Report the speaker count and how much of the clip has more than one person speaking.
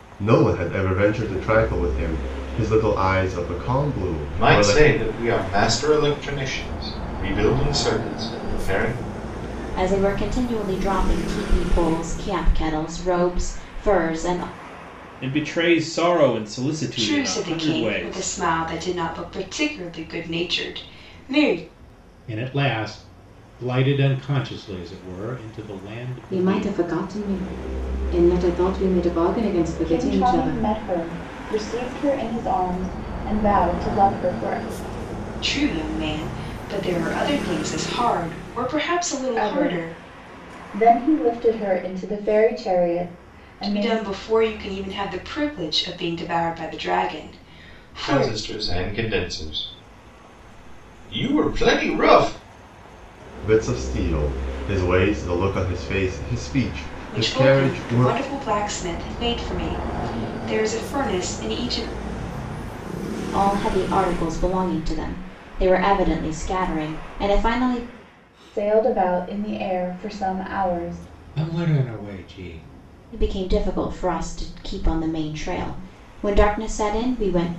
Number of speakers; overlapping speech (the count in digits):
8, about 8%